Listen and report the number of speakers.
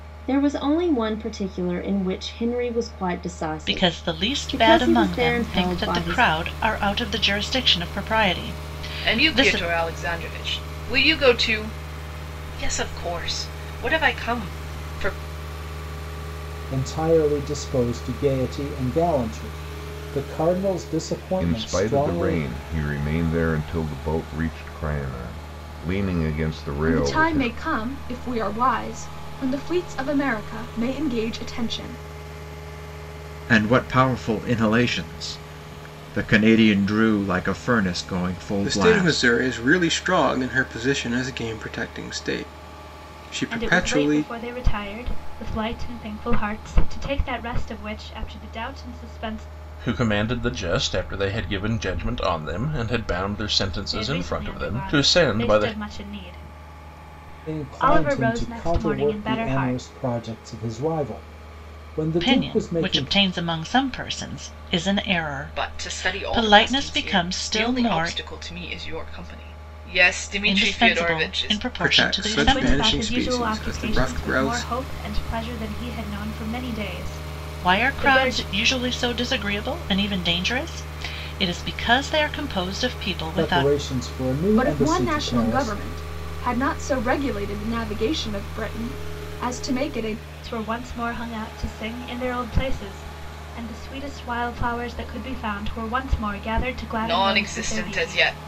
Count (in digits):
10